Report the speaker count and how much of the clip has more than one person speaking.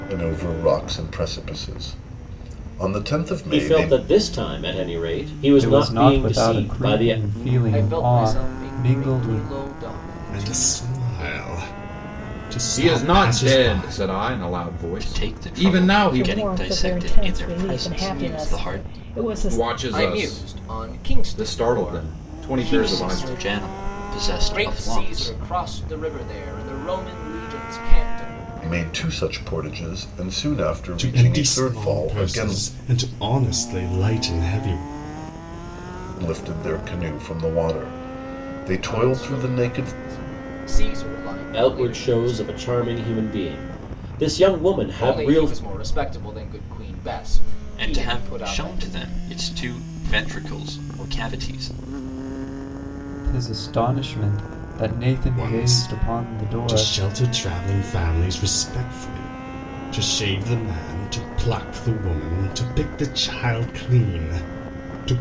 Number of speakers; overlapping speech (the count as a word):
eight, about 34%